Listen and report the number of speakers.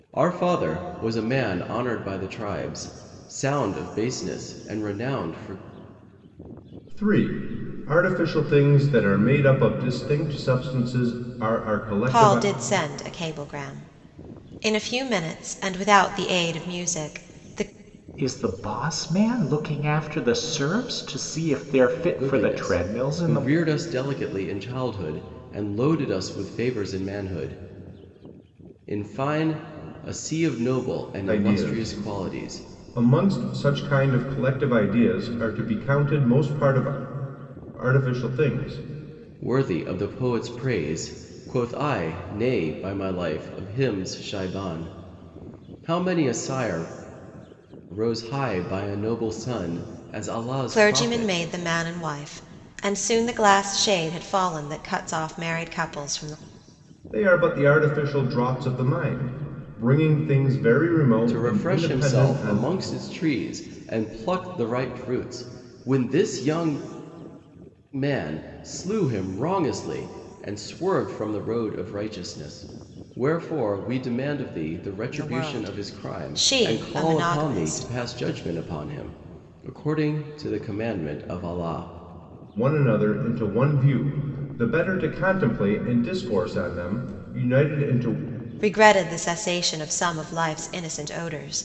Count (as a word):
four